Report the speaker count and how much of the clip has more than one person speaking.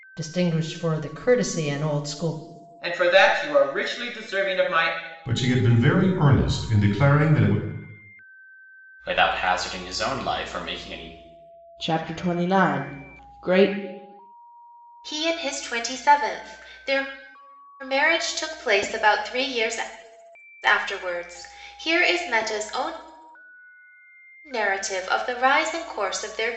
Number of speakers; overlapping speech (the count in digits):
6, no overlap